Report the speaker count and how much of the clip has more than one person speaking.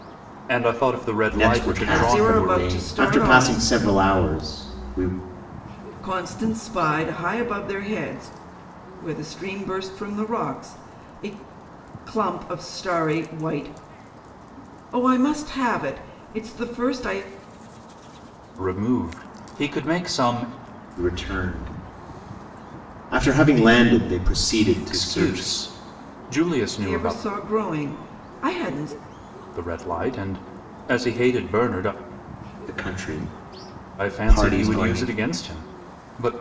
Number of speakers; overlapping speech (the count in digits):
3, about 12%